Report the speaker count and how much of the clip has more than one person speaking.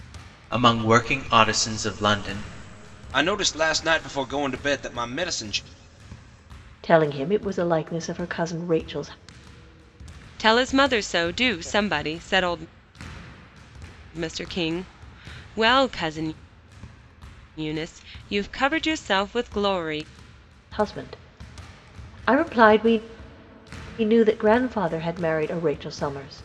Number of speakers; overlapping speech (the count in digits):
4, no overlap